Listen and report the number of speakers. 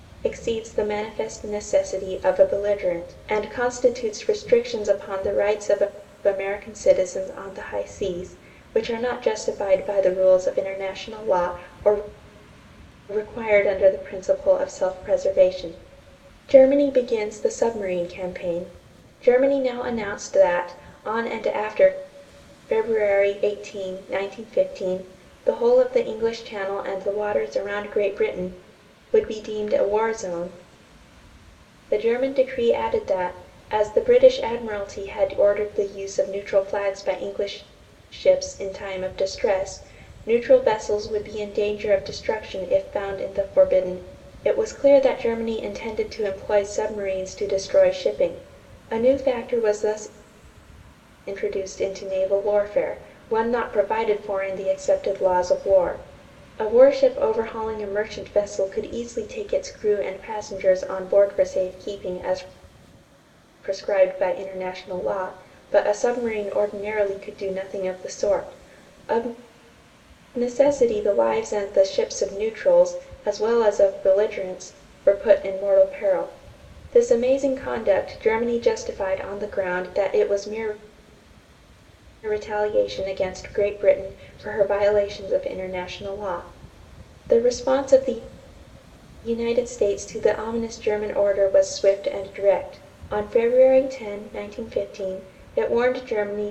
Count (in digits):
1